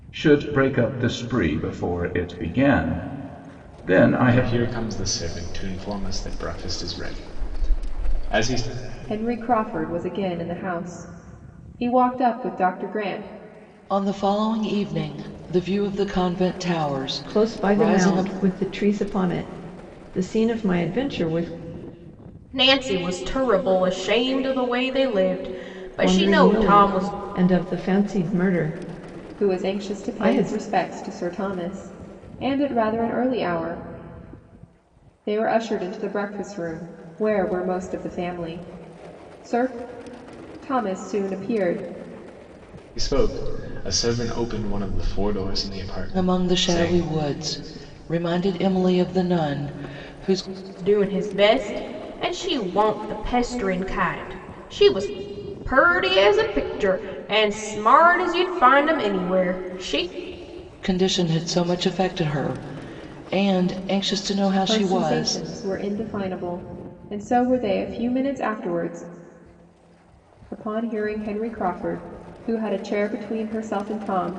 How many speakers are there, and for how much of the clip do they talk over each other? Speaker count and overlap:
6, about 8%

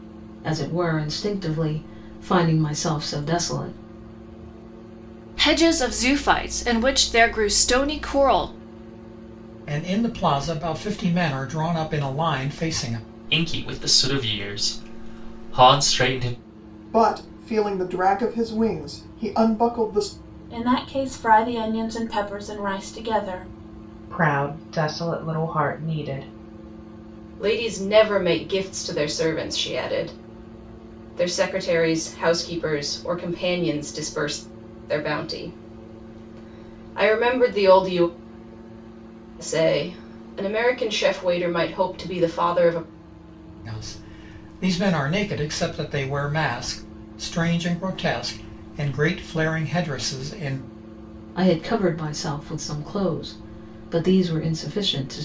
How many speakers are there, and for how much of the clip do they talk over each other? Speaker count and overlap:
8, no overlap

